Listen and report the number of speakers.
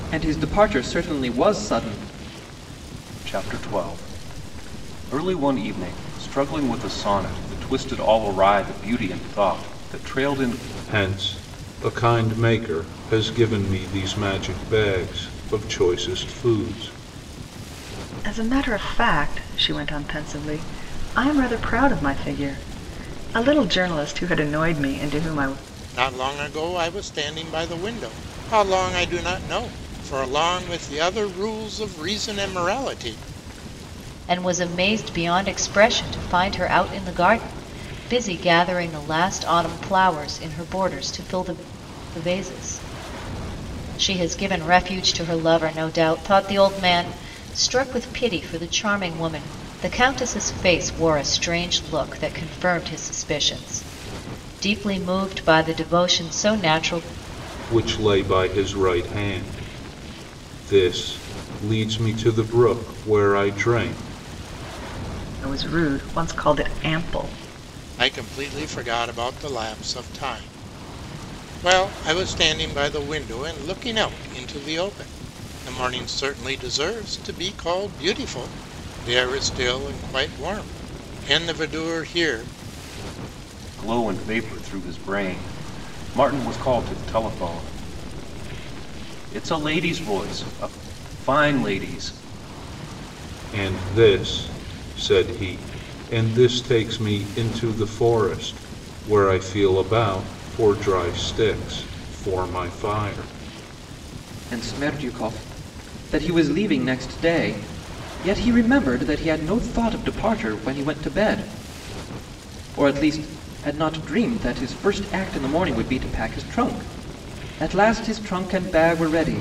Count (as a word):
six